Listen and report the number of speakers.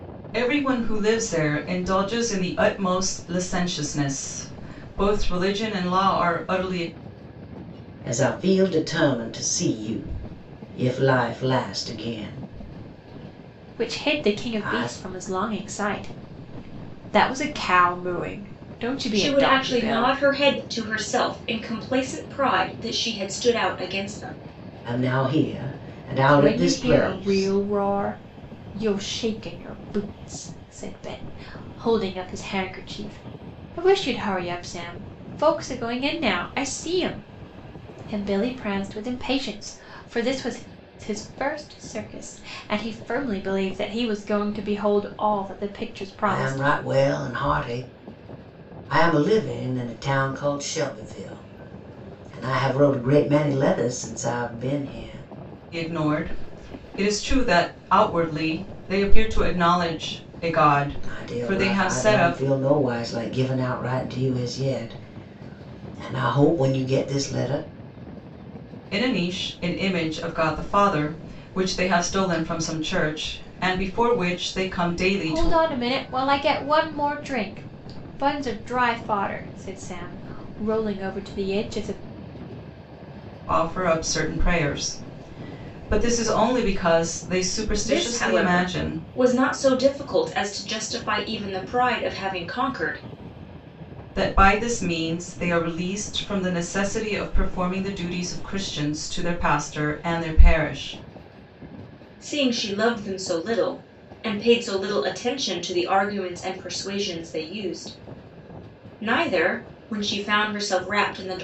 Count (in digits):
4